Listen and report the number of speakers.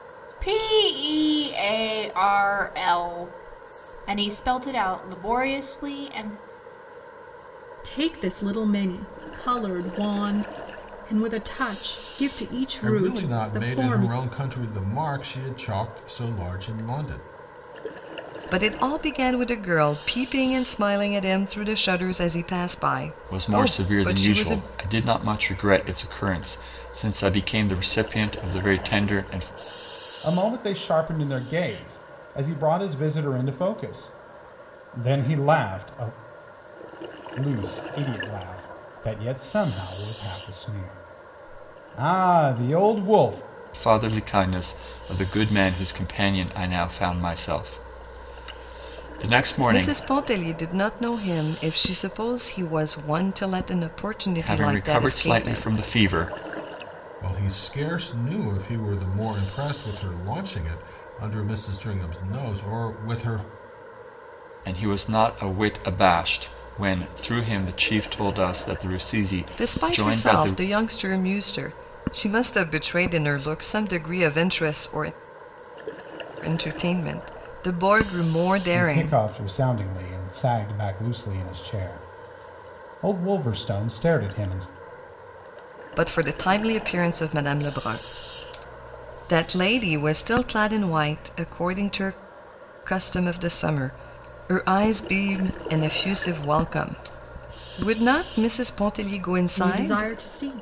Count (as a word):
six